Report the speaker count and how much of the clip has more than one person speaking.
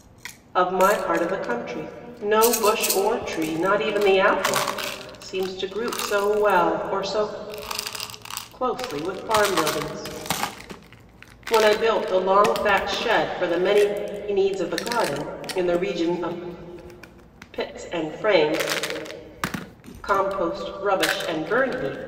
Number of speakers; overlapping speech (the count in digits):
1, no overlap